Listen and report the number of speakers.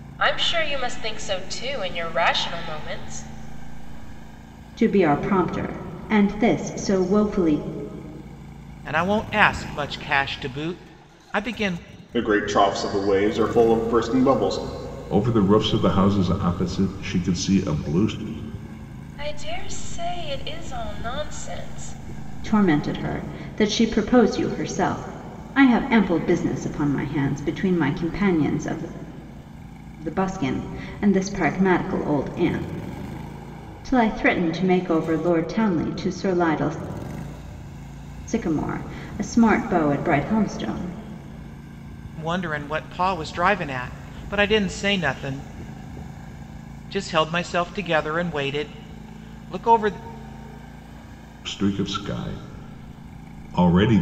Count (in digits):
5